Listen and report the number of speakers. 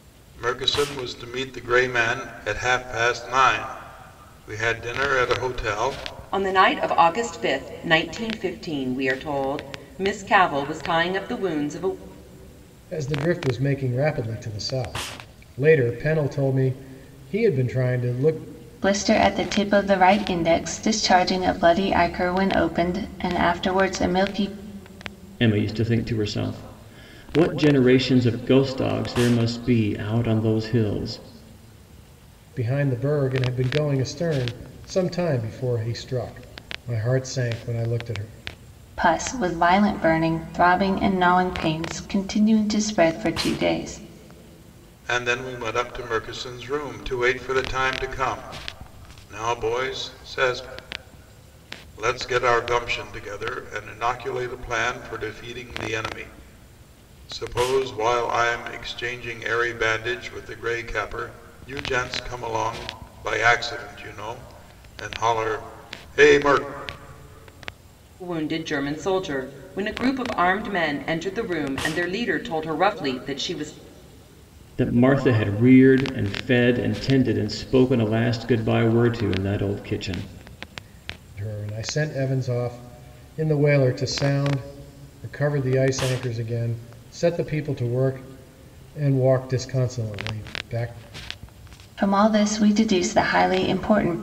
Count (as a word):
five